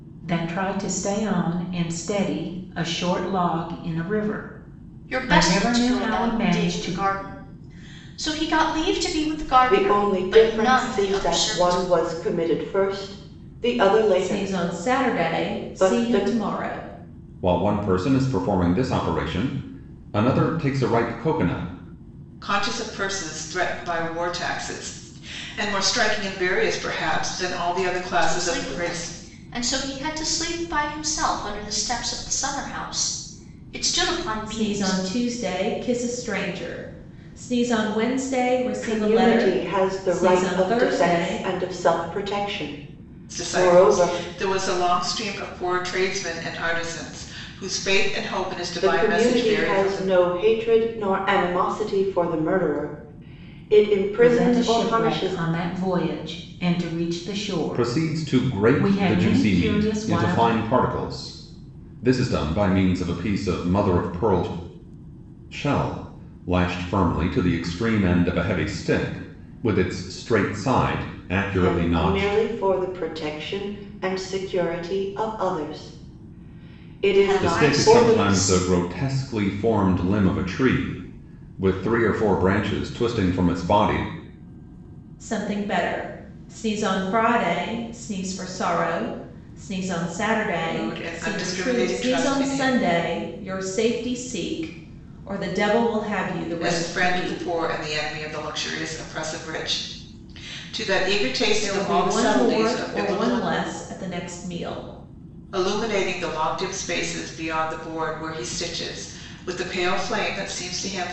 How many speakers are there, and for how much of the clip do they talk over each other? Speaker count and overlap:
6, about 22%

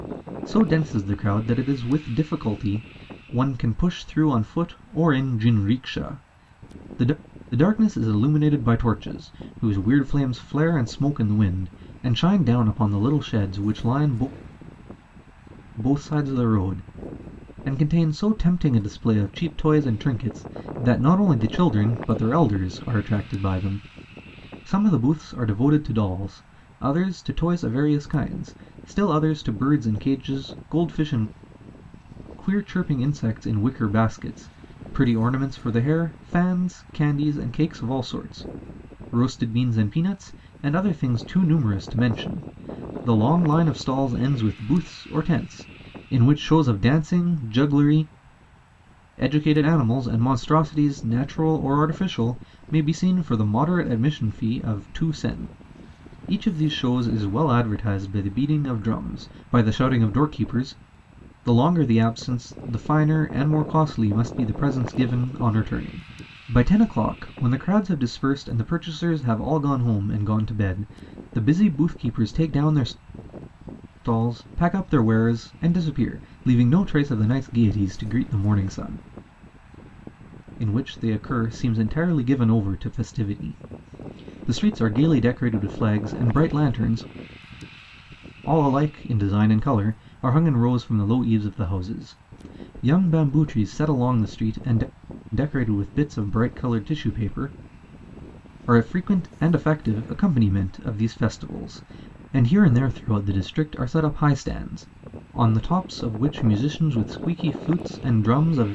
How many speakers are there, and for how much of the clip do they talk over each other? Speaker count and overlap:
1, no overlap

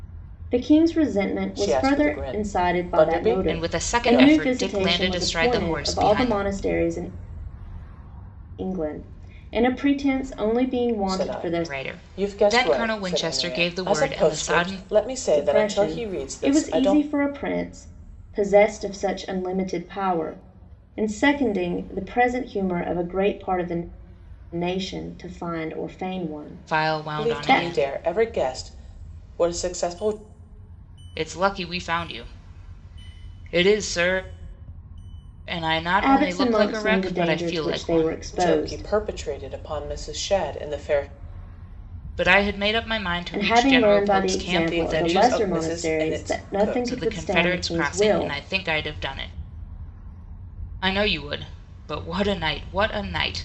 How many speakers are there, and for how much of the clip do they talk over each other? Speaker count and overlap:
3, about 37%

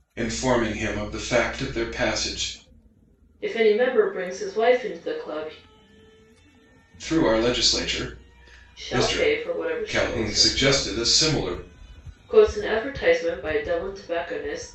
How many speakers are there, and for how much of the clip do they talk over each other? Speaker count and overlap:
2, about 12%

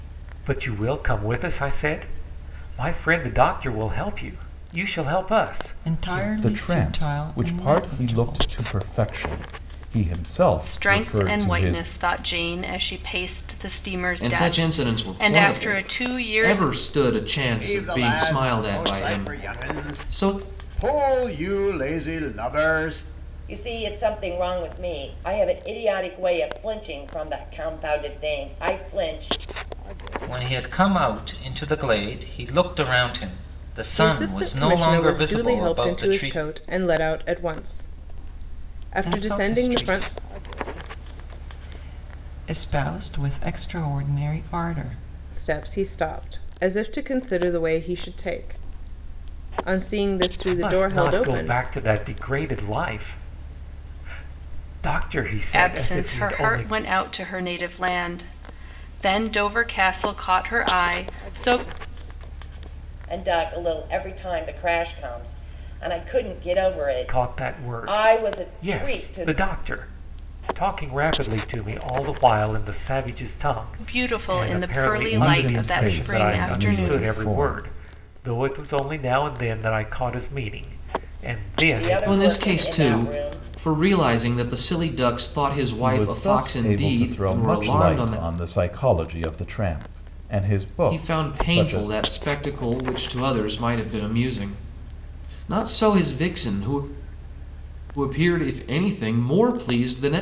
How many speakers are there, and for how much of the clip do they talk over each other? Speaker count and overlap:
9, about 27%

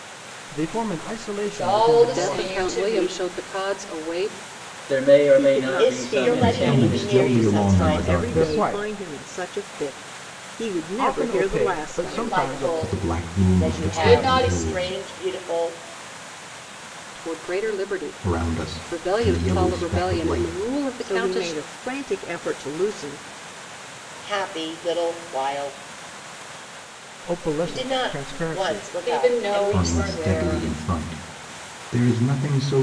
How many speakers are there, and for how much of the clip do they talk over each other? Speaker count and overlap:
7, about 47%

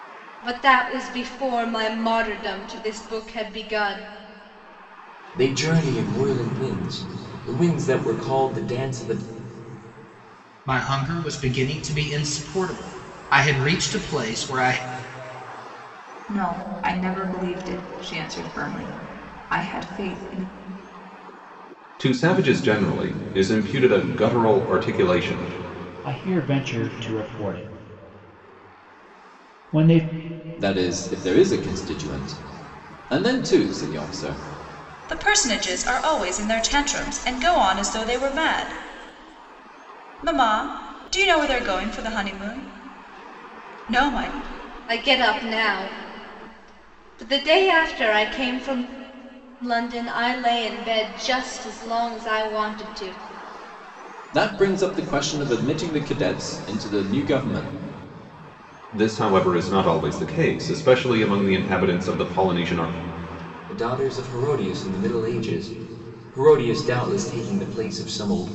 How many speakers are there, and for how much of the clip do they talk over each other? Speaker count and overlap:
8, no overlap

